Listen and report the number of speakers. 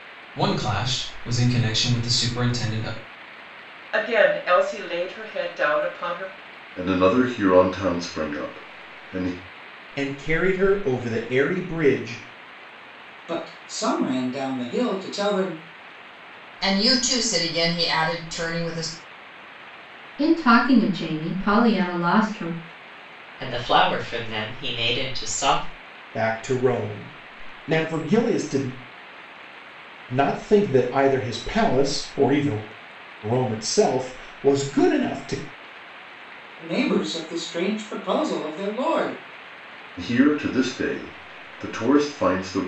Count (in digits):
8